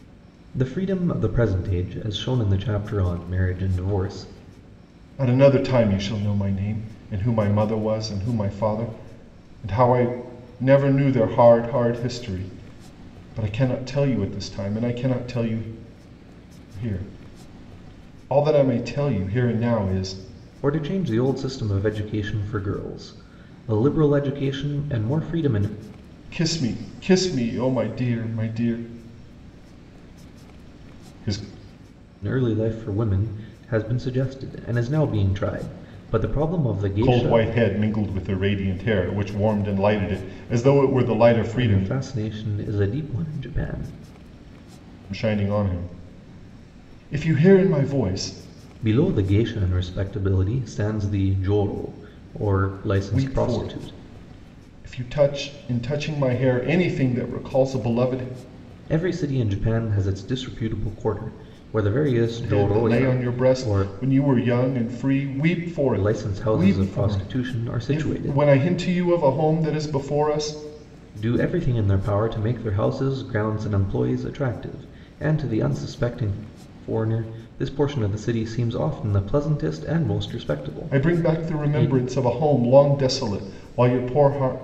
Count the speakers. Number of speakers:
2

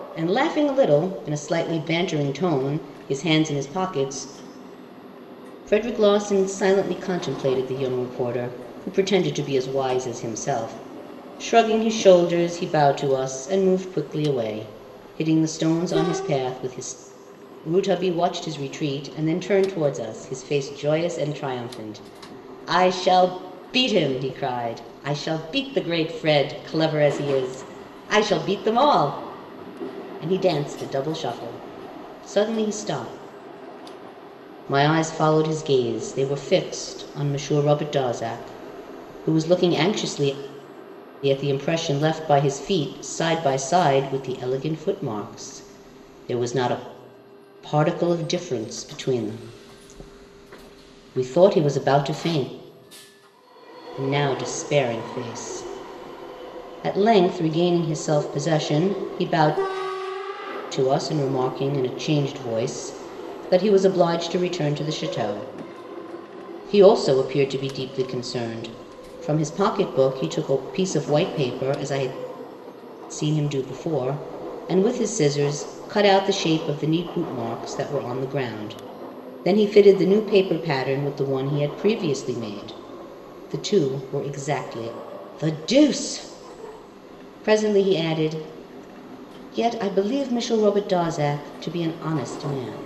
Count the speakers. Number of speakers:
1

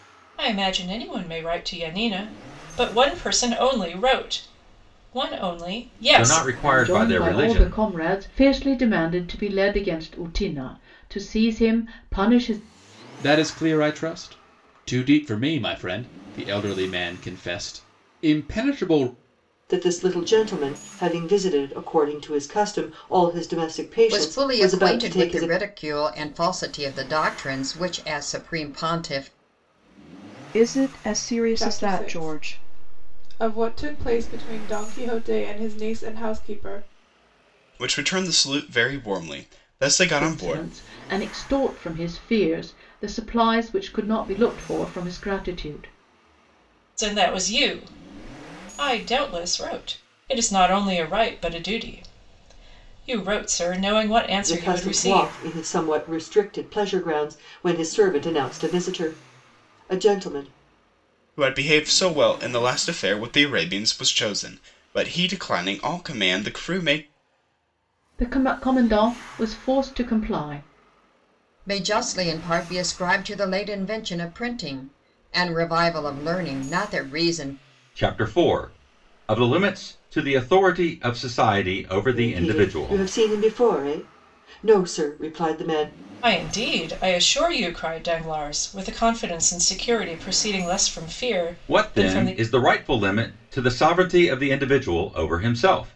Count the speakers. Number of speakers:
9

